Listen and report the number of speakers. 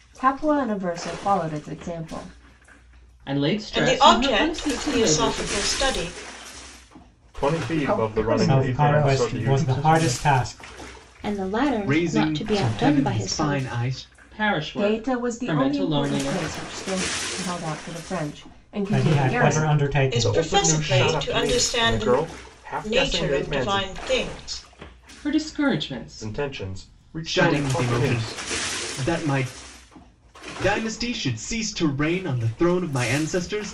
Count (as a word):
eight